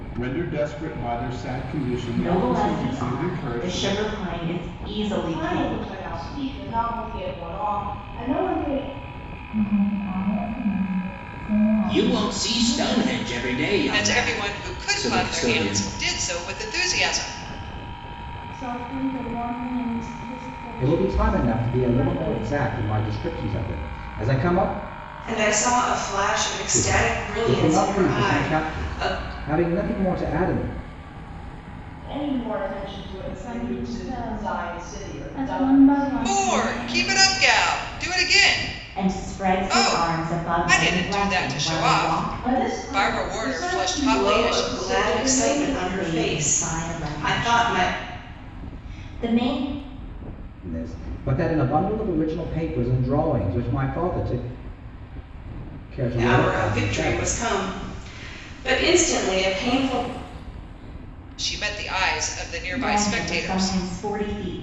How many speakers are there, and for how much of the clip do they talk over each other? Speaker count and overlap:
nine, about 38%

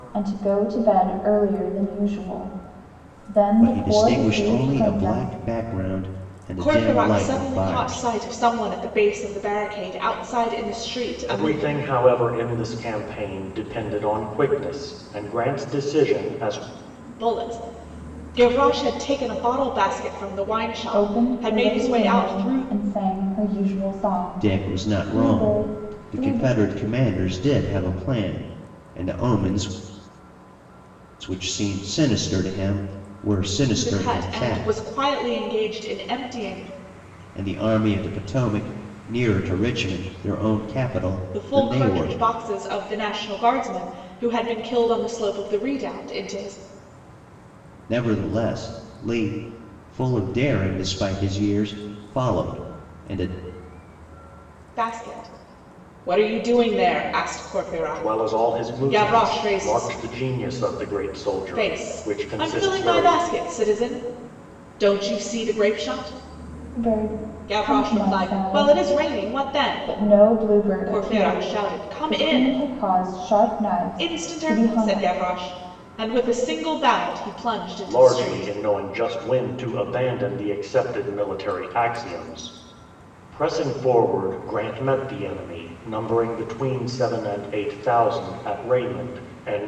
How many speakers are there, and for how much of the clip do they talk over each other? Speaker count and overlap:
four, about 22%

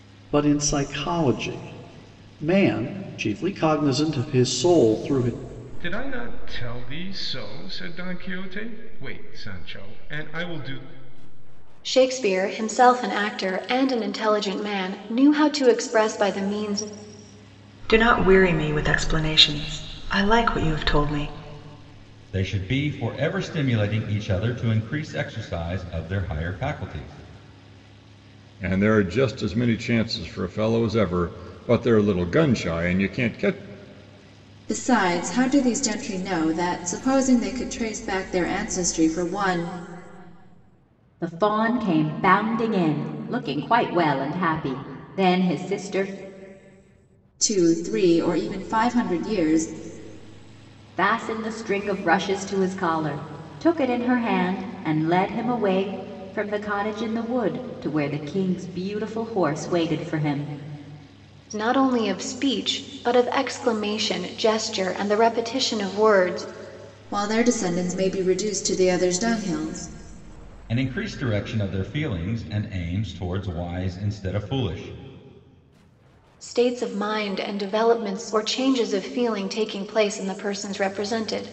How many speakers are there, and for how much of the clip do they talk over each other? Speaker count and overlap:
eight, no overlap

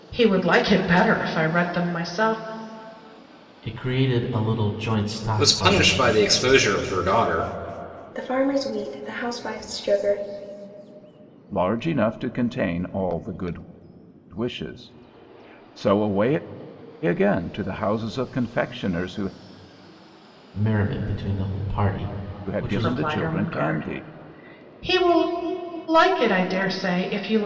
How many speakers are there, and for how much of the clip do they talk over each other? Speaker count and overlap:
five, about 8%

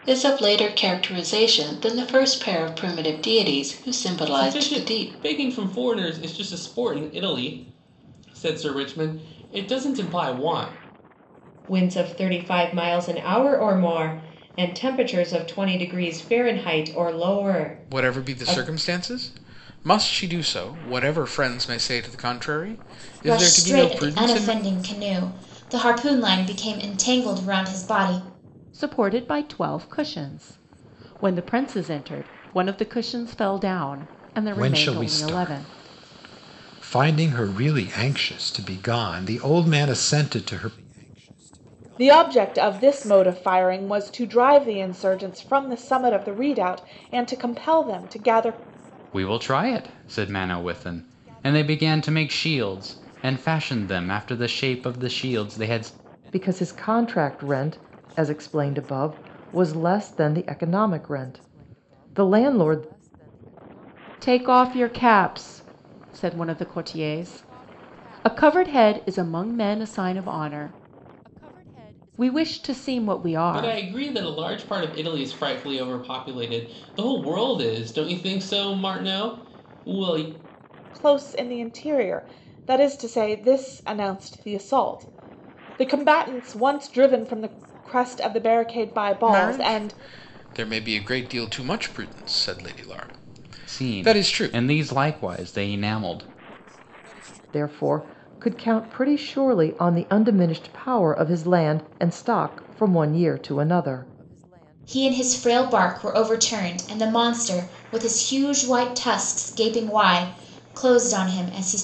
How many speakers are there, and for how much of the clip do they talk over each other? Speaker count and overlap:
ten, about 6%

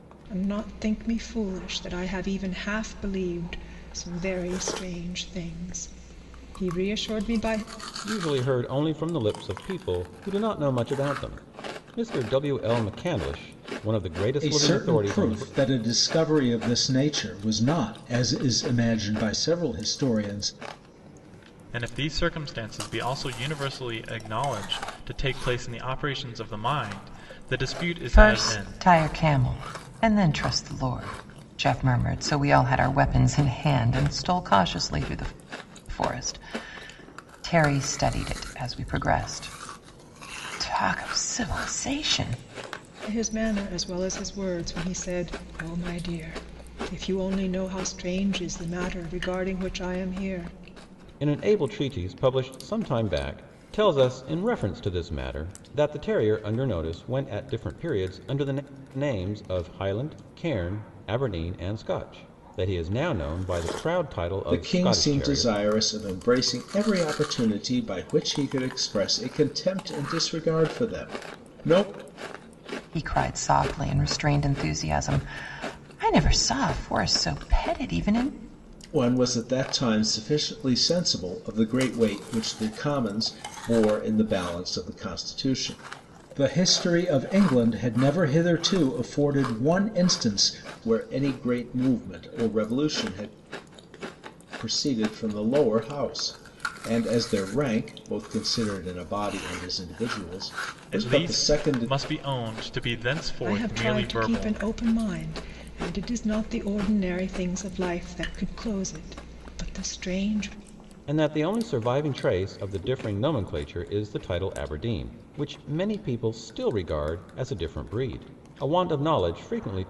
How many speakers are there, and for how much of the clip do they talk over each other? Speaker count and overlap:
five, about 4%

